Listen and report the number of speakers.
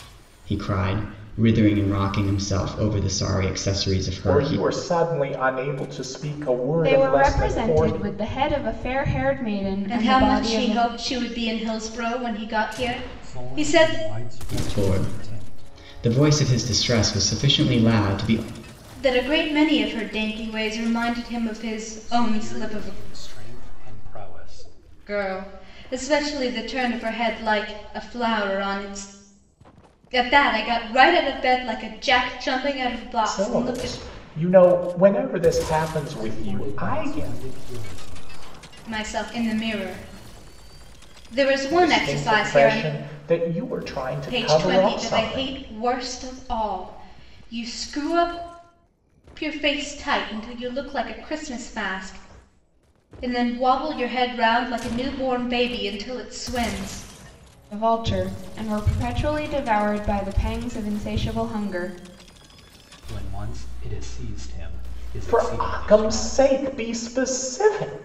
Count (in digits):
5